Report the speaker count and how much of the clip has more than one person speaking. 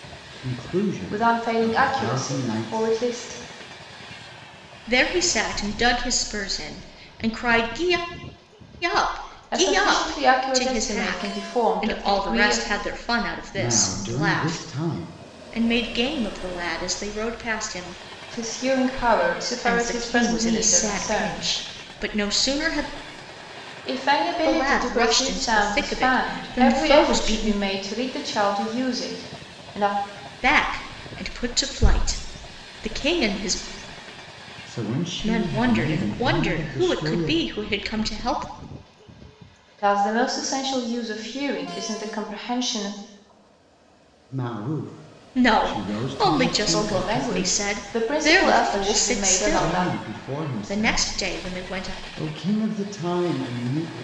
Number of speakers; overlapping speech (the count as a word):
three, about 38%